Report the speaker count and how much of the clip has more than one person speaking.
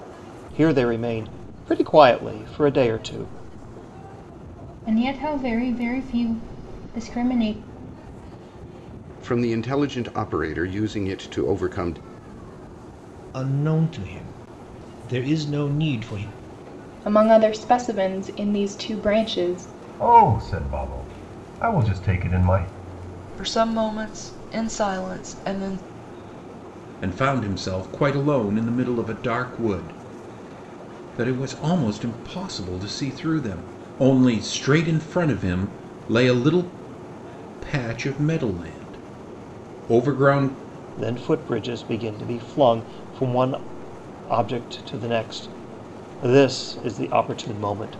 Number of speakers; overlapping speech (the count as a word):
eight, no overlap